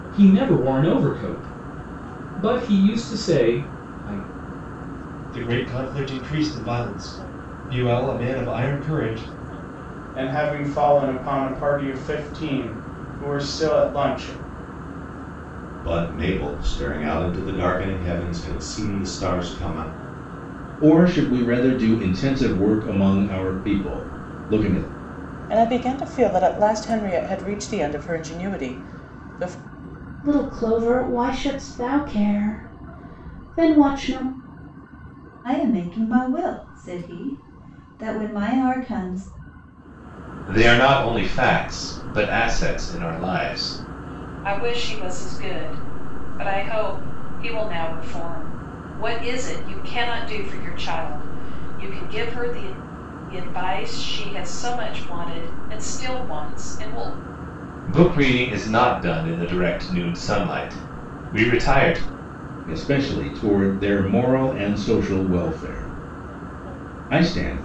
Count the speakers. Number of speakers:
10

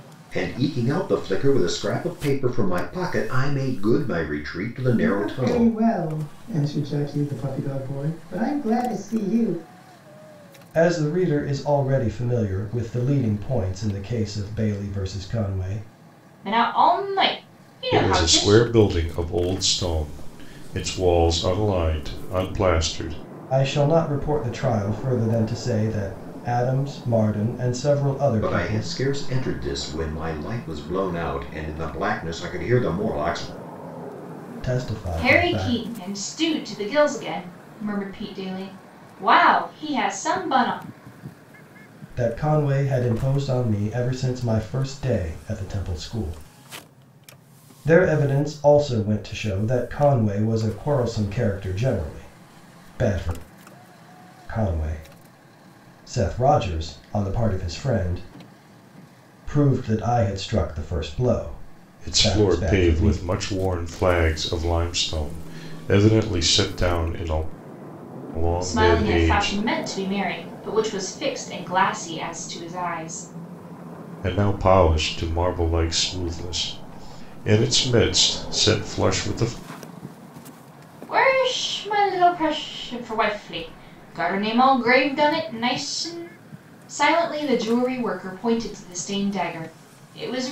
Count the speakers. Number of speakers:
5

